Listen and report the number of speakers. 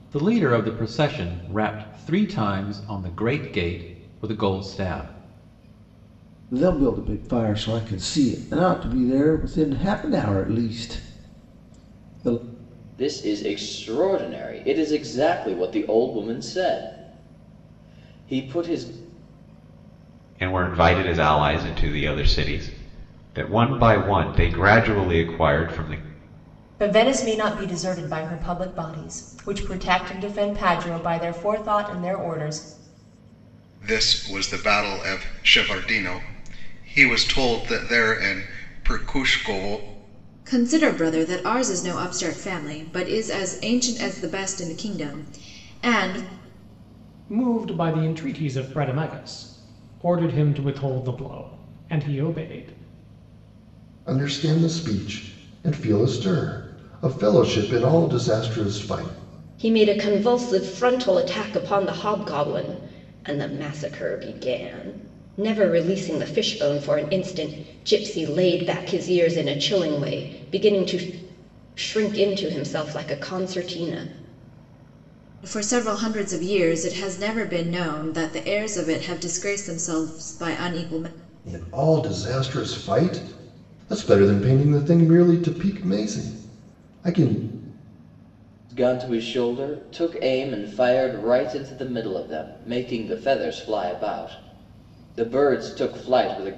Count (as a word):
ten